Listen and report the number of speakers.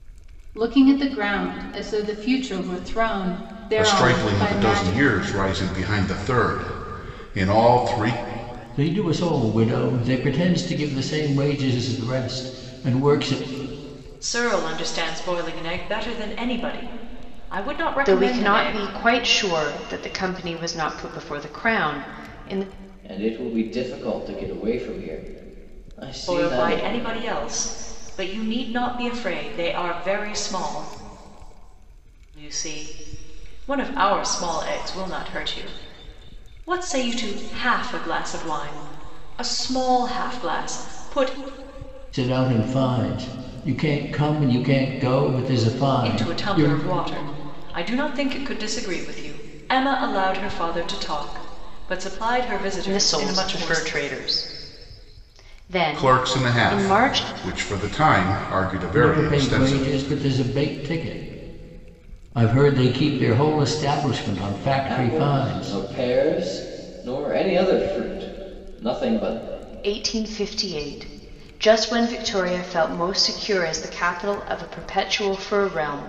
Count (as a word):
six